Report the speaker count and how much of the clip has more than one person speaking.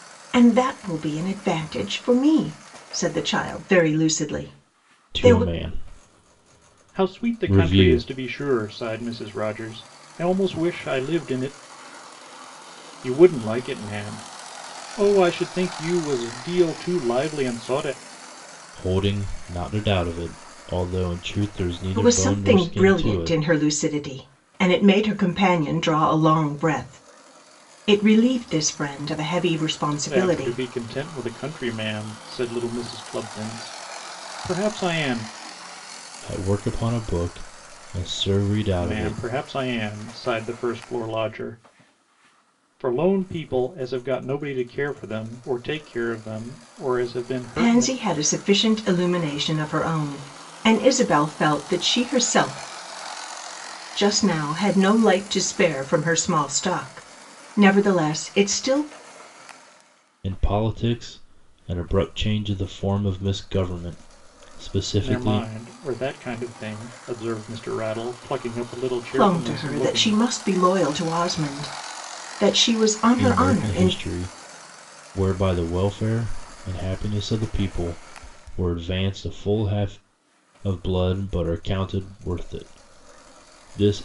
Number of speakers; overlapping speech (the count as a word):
three, about 8%